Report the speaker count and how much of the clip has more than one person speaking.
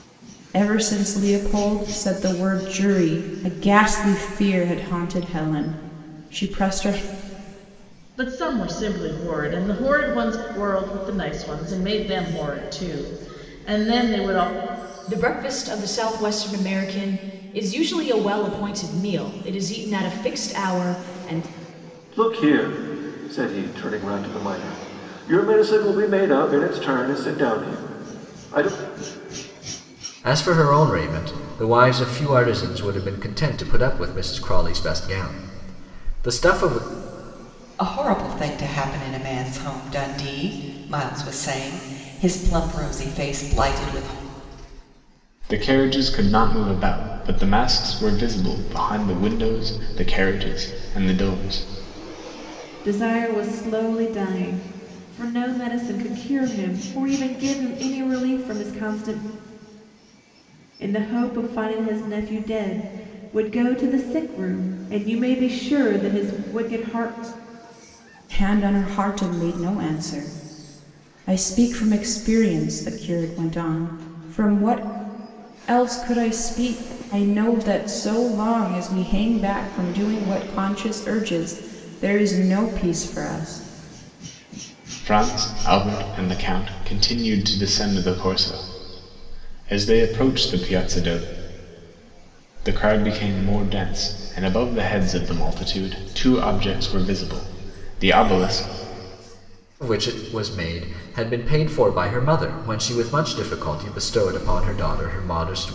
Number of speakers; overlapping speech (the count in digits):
8, no overlap